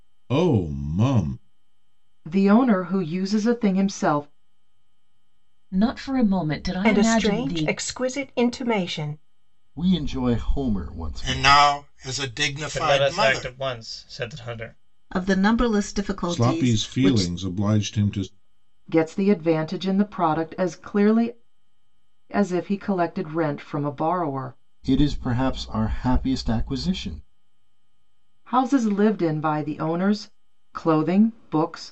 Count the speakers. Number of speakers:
8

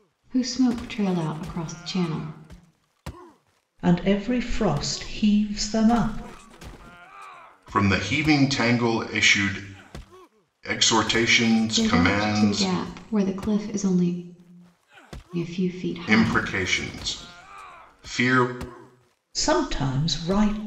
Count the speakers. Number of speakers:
3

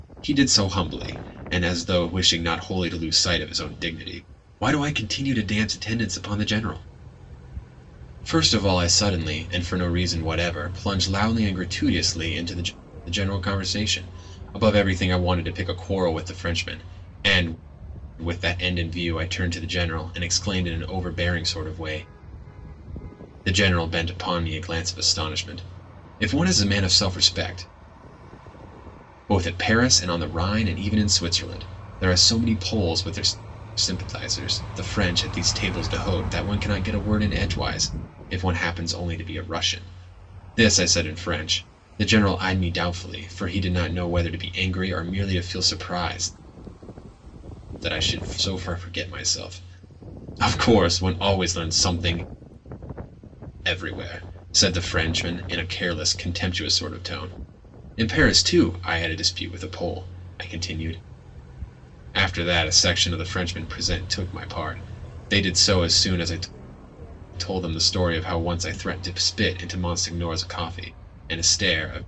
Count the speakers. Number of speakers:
1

